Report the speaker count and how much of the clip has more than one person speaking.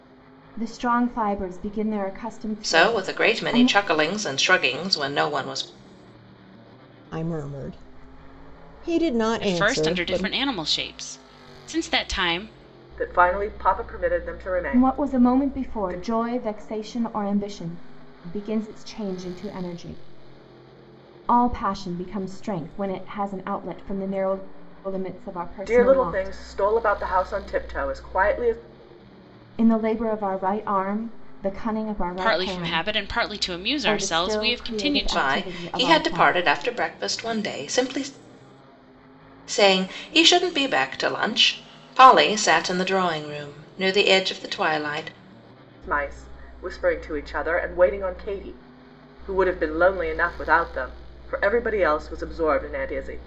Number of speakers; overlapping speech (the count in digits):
5, about 14%